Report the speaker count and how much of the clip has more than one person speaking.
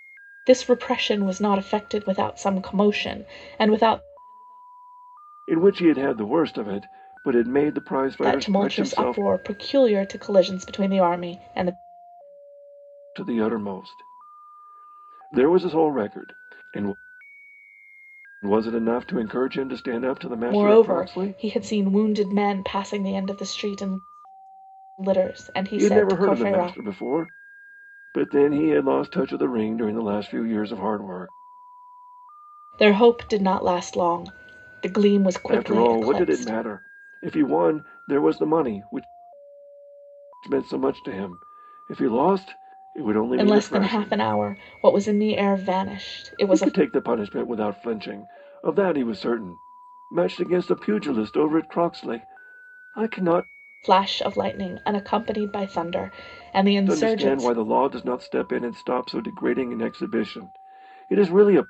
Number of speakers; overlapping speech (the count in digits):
2, about 10%